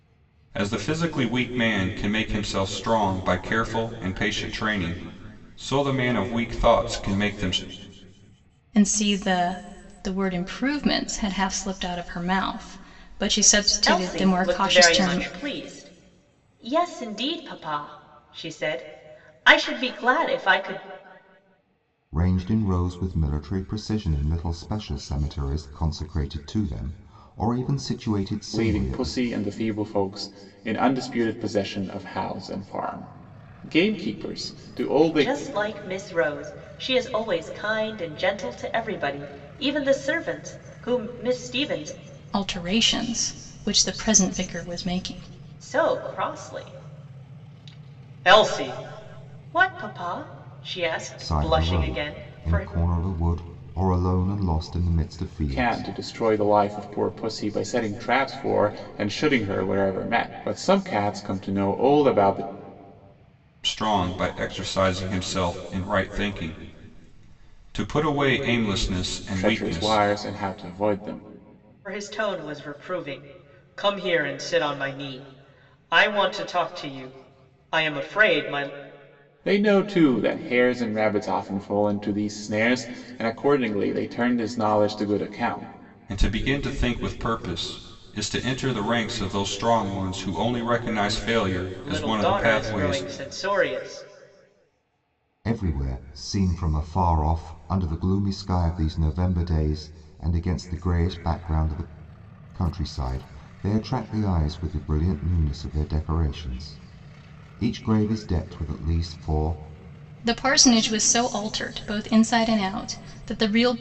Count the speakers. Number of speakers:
5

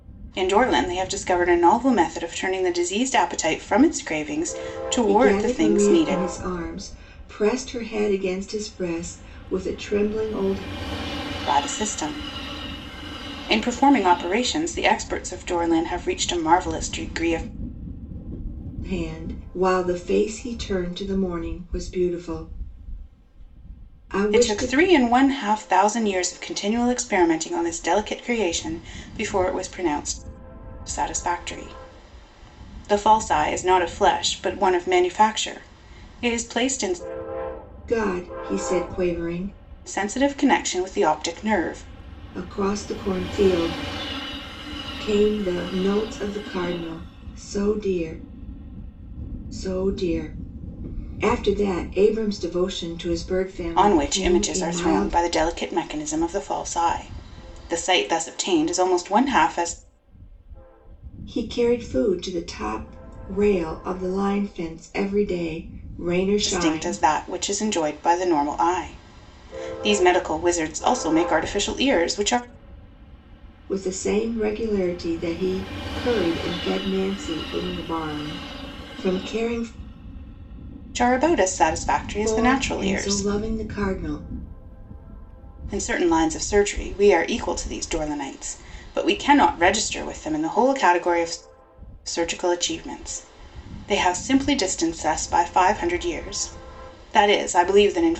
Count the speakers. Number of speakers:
2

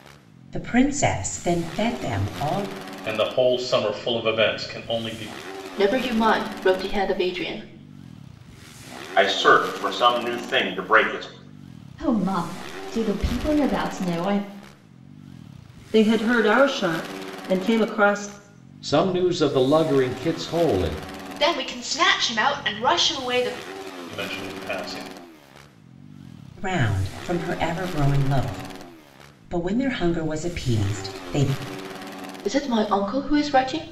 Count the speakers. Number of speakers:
8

